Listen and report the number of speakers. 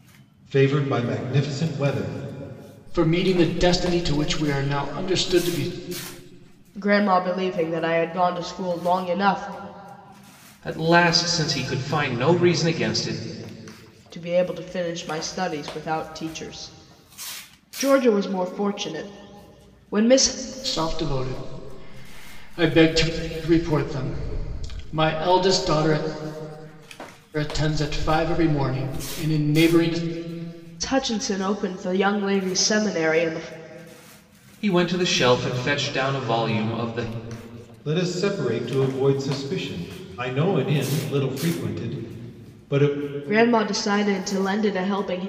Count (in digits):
4